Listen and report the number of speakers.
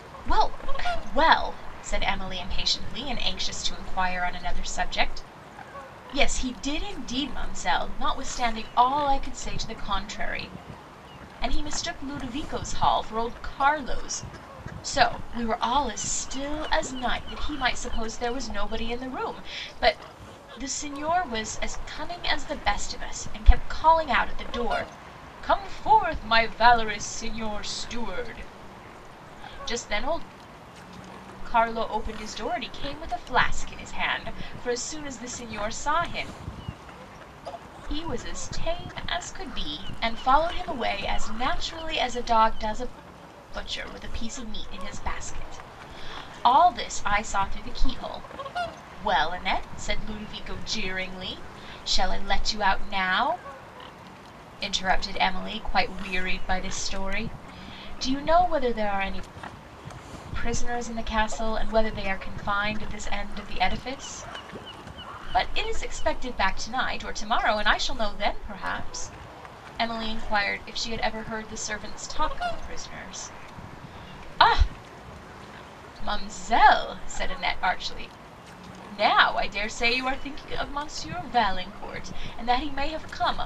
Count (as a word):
one